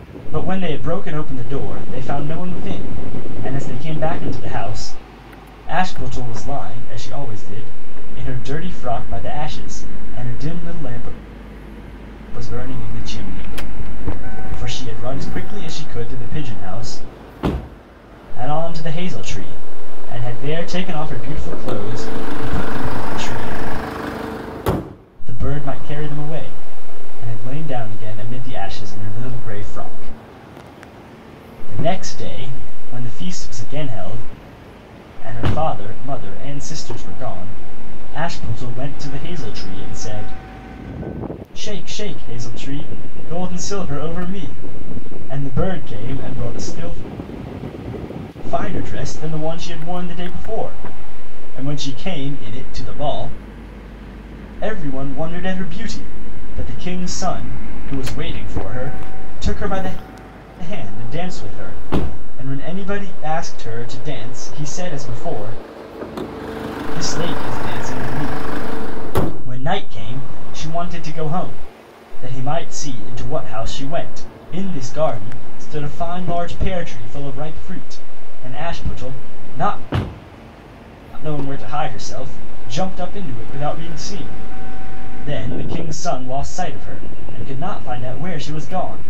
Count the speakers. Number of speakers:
one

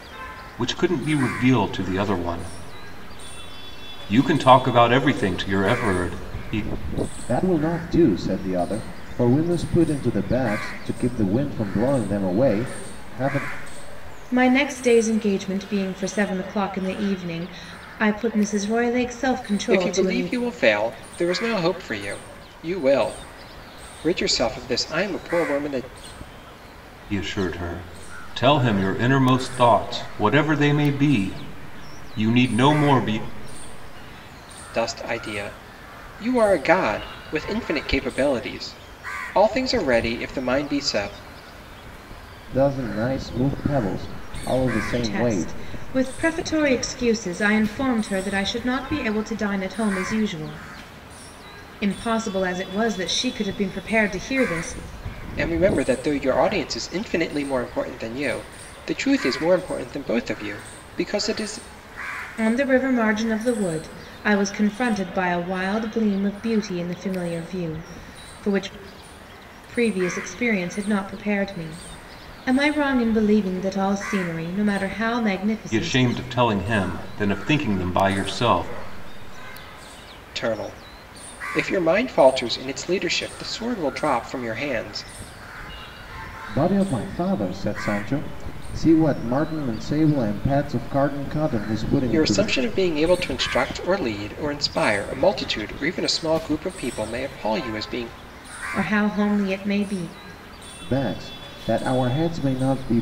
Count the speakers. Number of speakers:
four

